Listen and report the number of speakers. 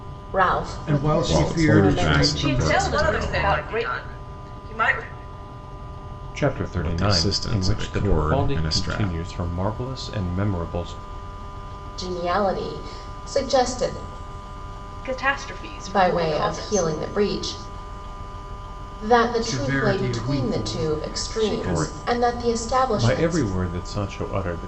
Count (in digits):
6